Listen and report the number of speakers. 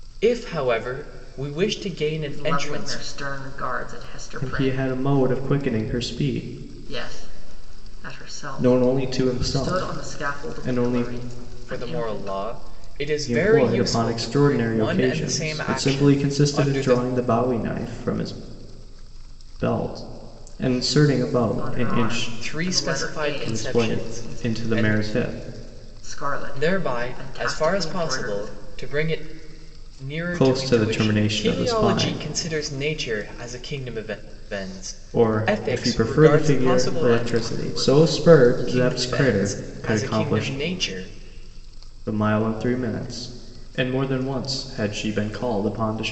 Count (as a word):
three